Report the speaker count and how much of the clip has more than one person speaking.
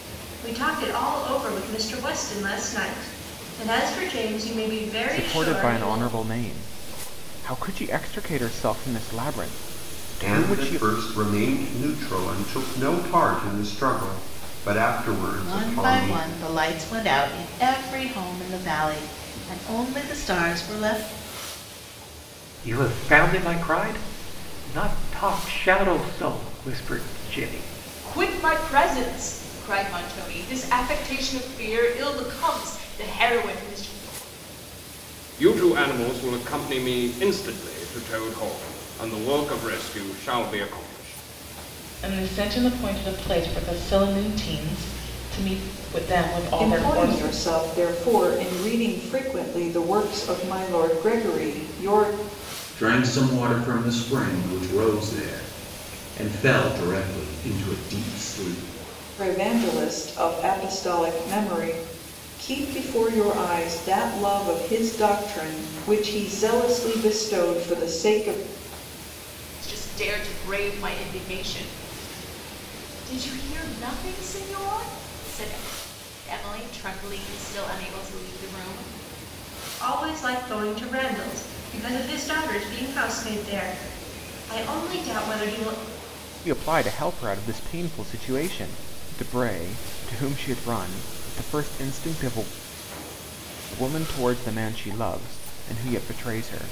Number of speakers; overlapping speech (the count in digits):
10, about 3%